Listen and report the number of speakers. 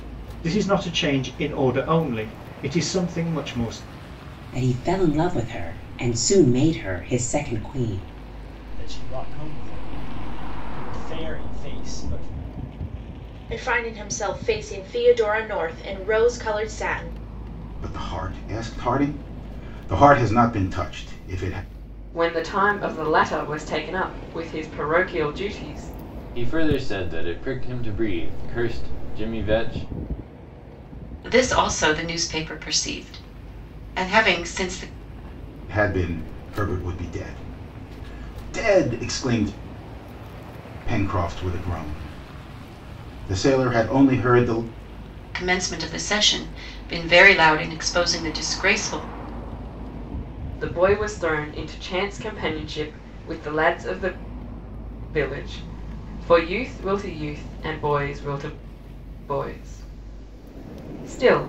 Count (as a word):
eight